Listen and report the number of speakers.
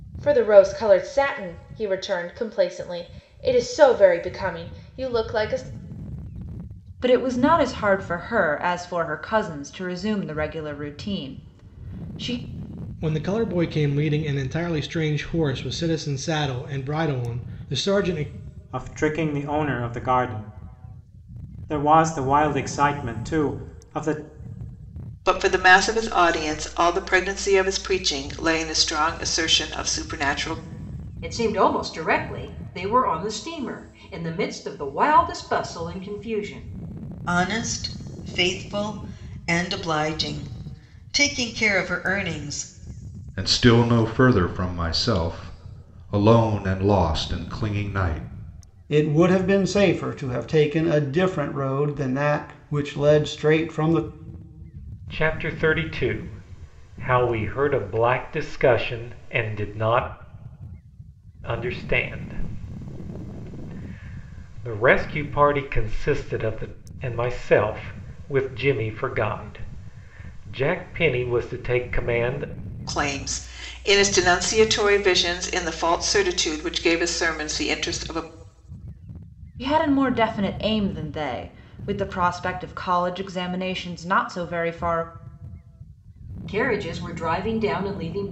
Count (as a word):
ten